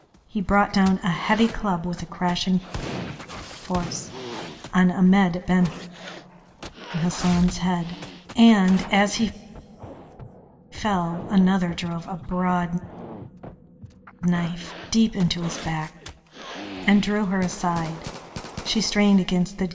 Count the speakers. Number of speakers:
one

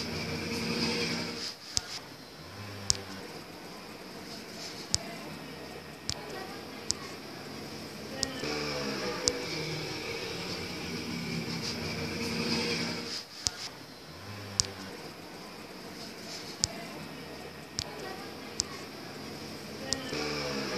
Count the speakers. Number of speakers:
zero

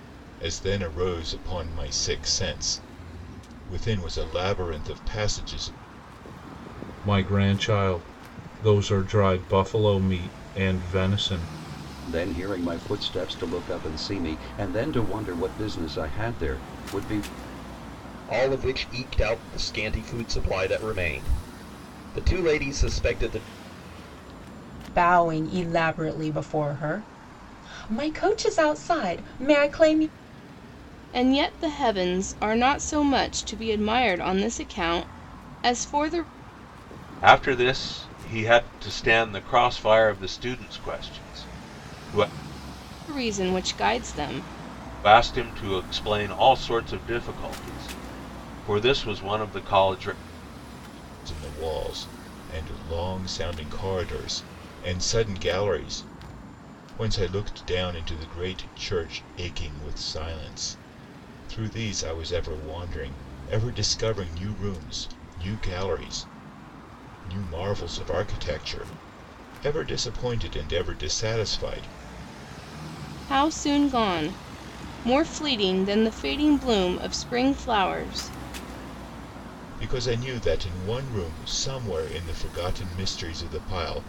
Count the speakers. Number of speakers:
seven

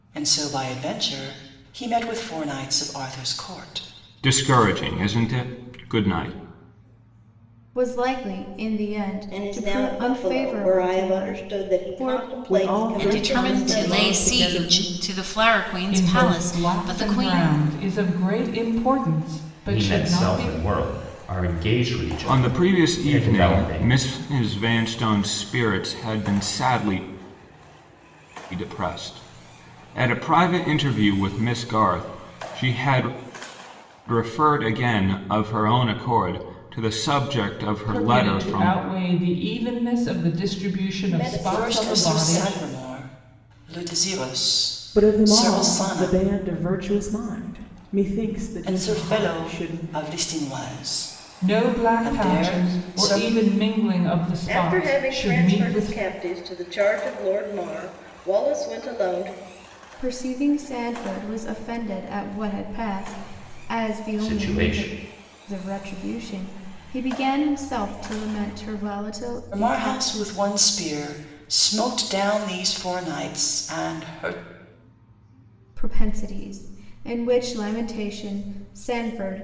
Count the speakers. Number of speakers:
eight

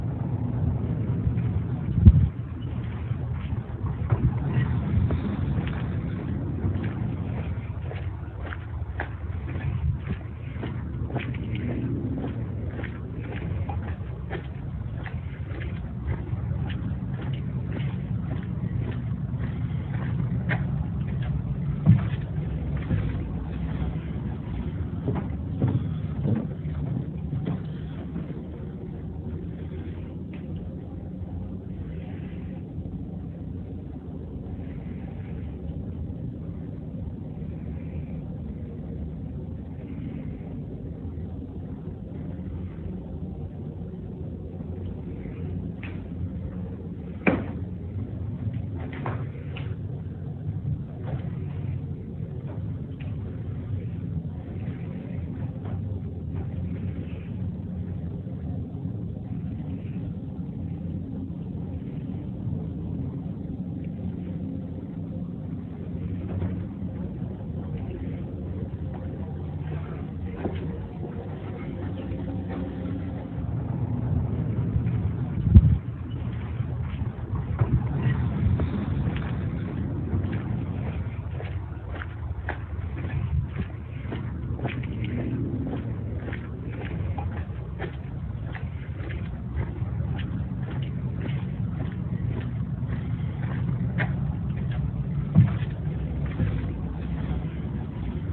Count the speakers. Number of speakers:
zero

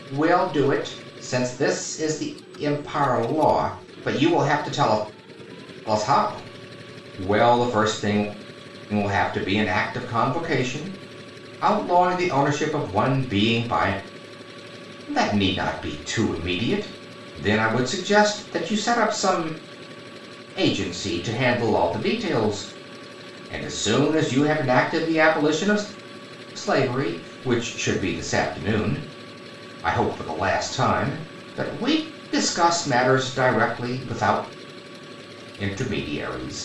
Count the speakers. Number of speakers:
one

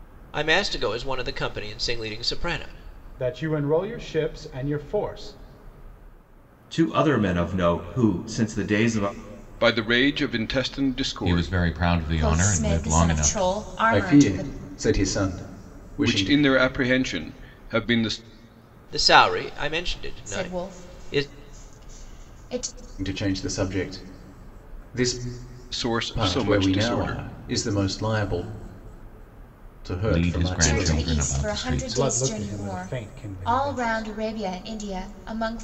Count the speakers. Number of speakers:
seven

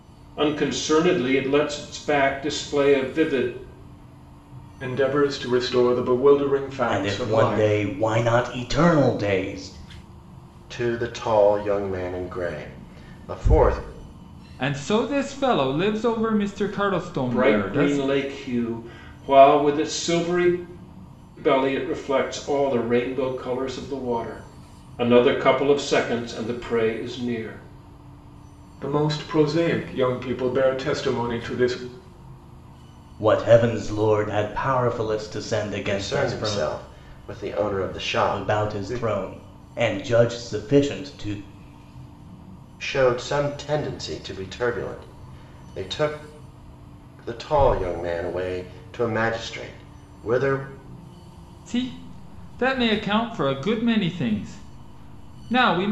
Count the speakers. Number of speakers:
five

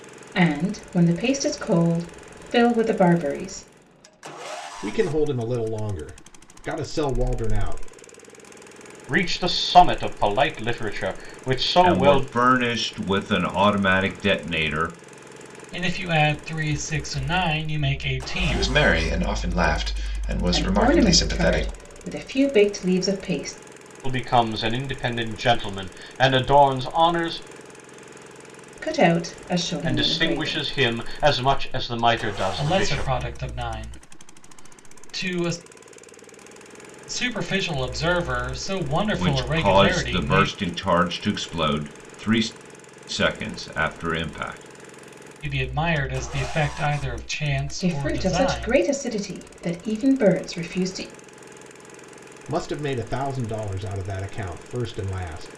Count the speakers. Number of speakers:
six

